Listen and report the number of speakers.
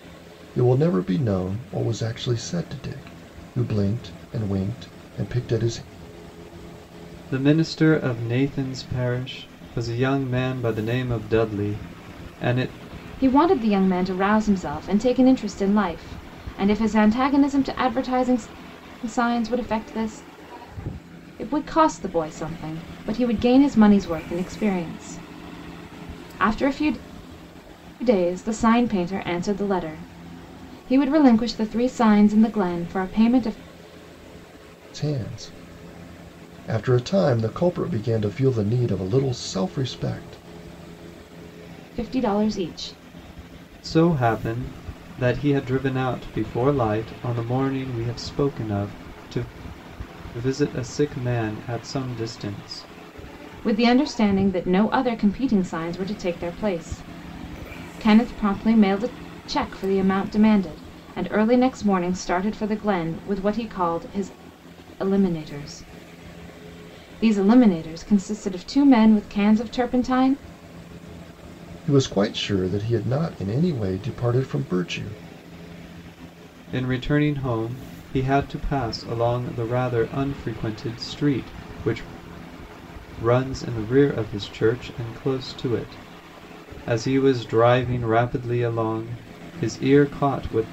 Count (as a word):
three